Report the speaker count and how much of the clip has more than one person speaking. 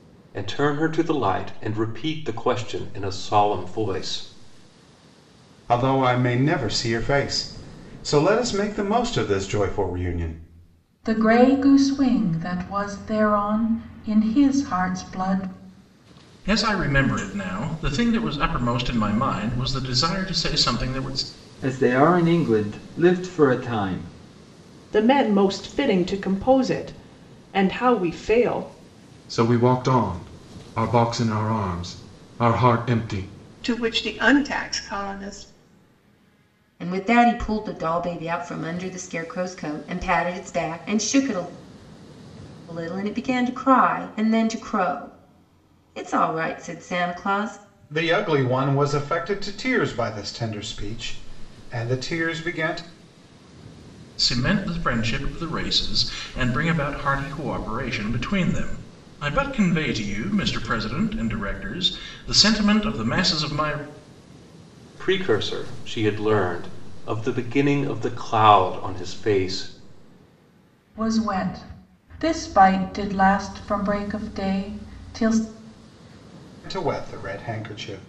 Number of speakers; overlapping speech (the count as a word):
nine, no overlap